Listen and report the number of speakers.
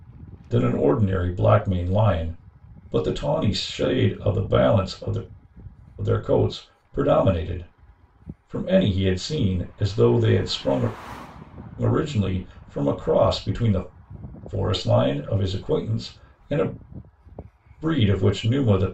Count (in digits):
1